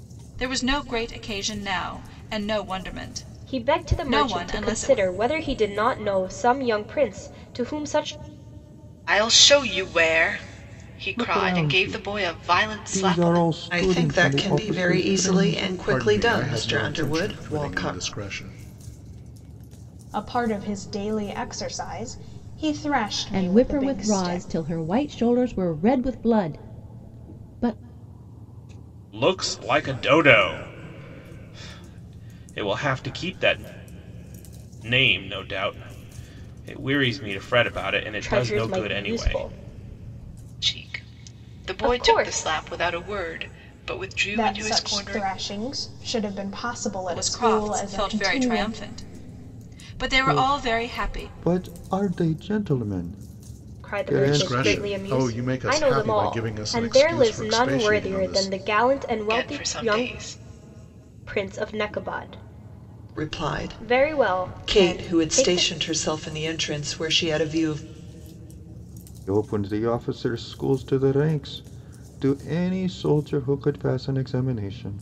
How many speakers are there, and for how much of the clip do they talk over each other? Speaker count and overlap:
9, about 33%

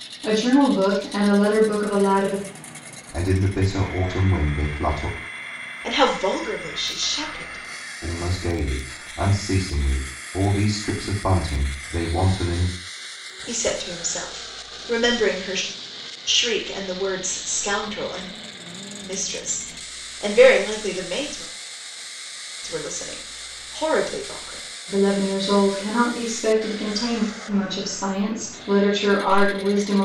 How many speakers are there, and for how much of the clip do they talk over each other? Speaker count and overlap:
3, no overlap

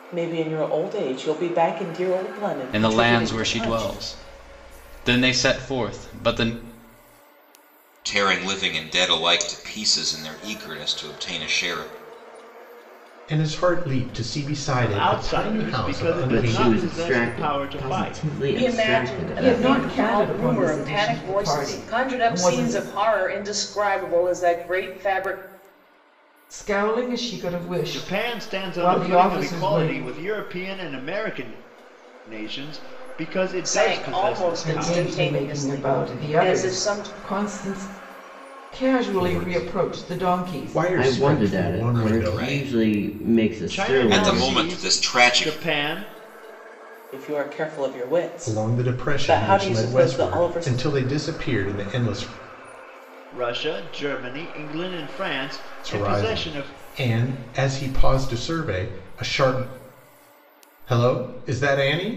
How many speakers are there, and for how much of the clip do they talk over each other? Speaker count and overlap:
8, about 39%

